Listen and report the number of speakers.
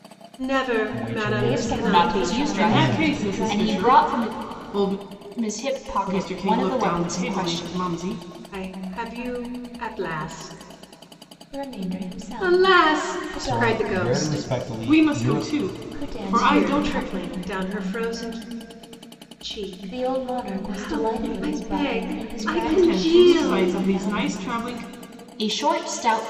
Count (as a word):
five